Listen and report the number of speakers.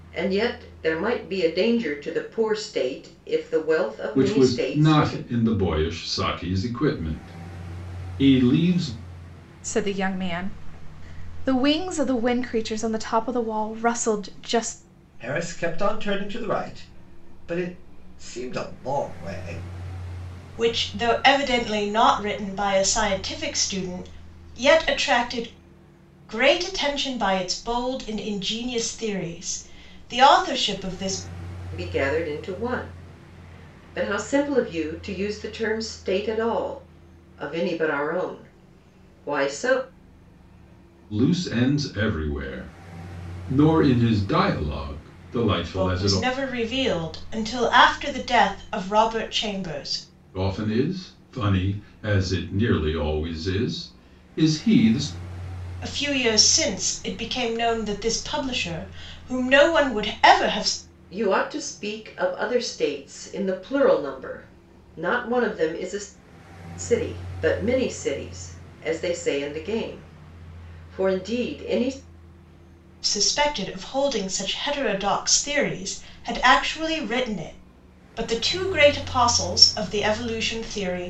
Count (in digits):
5